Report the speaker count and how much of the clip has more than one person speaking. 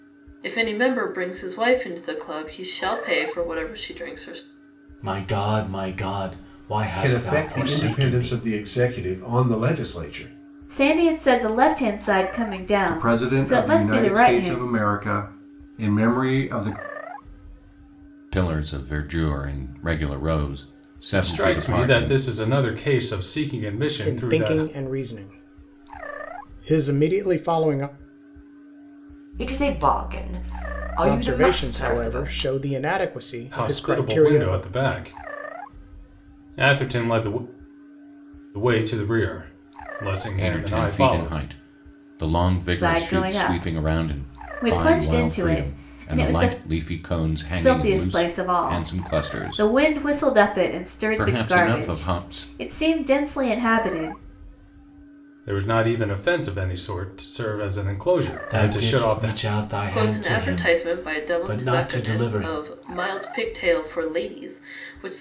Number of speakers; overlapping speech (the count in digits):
9, about 32%